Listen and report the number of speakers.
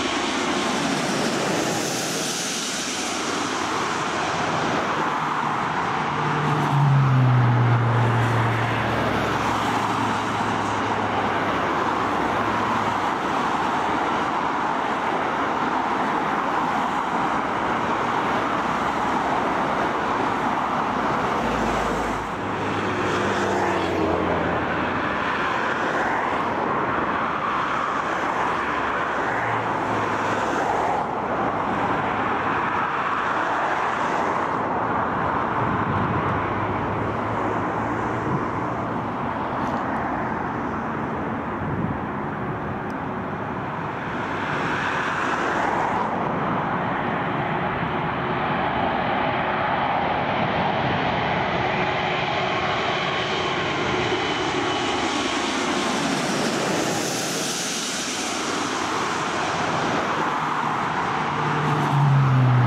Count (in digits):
0